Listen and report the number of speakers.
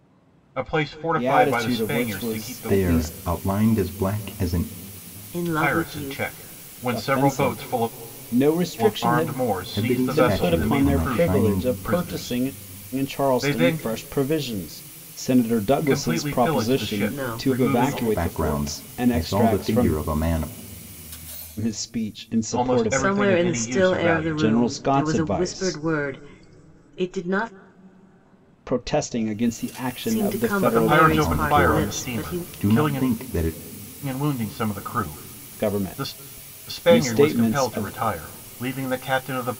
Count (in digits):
4